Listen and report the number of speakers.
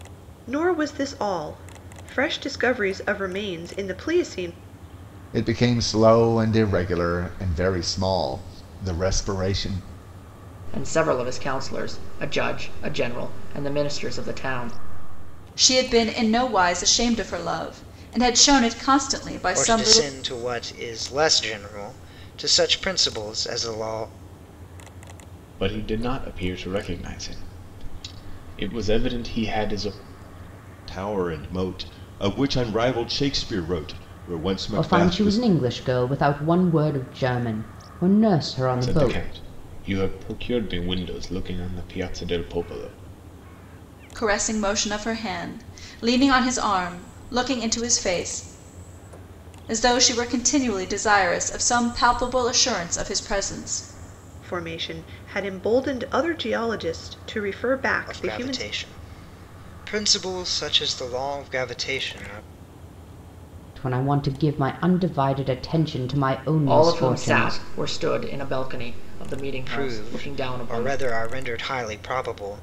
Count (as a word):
eight